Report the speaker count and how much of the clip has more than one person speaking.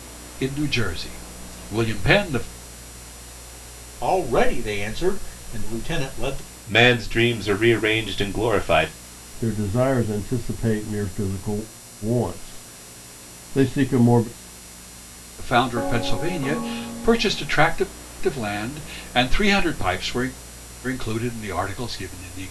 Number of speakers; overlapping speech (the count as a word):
four, no overlap